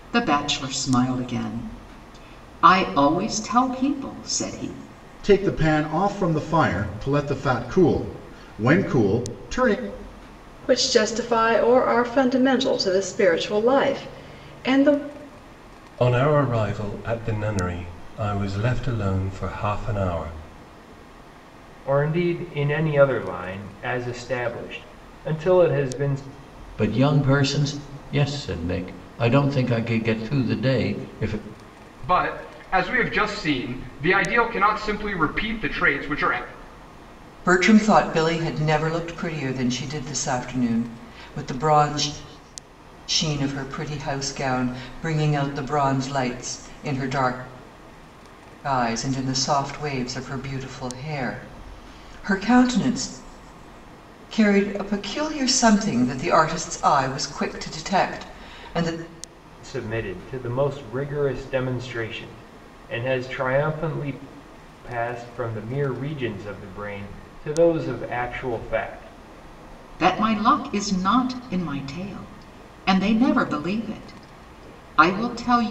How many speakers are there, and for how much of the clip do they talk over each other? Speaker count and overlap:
8, no overlap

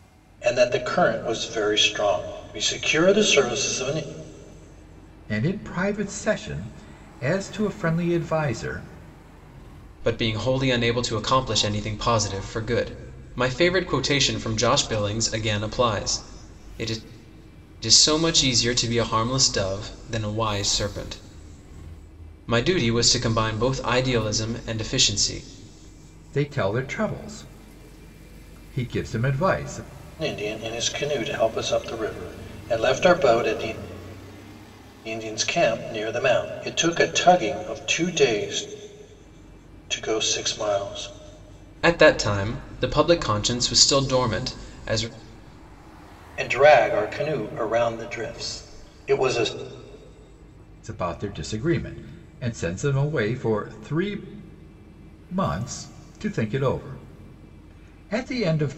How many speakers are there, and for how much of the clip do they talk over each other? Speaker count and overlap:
3, no overlap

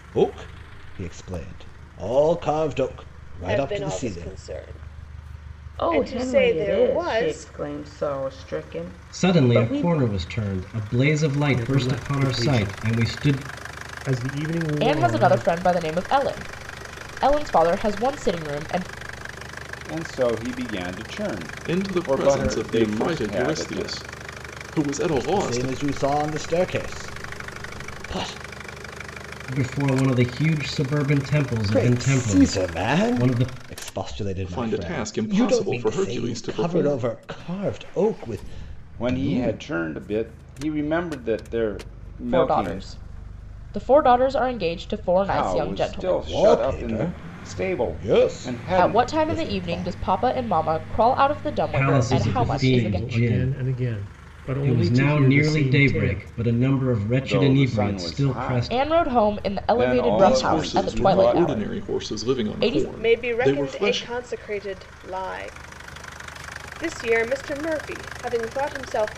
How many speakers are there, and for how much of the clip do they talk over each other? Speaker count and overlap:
8, about 44%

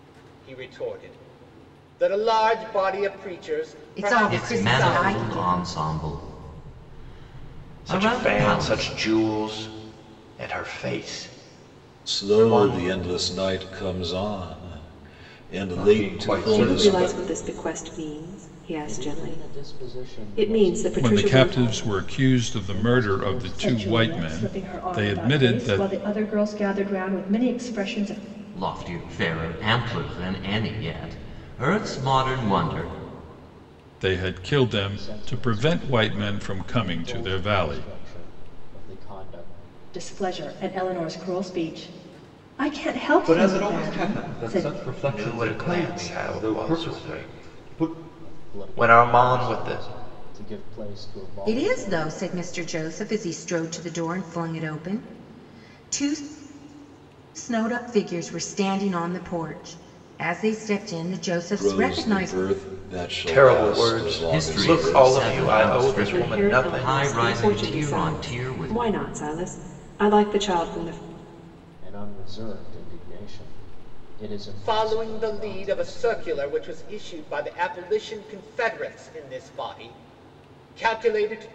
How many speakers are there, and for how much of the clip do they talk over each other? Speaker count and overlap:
10, about 38%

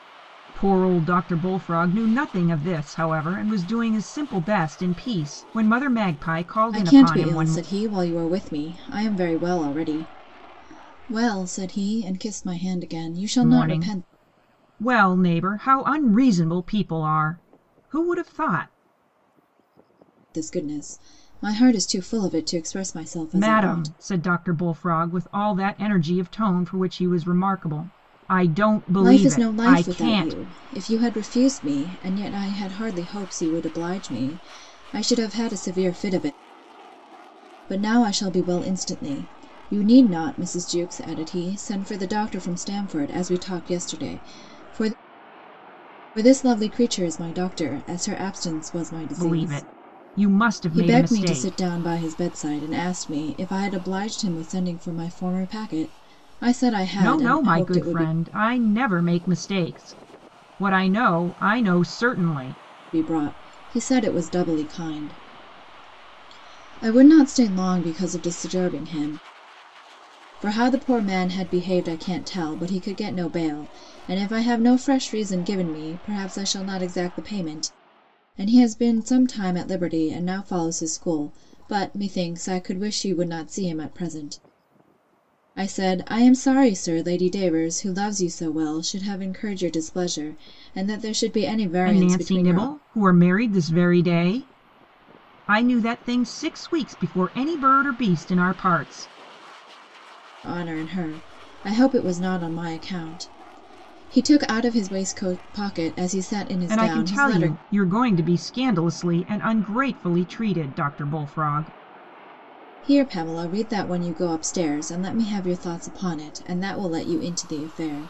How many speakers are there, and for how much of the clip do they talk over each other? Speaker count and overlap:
2, about 7%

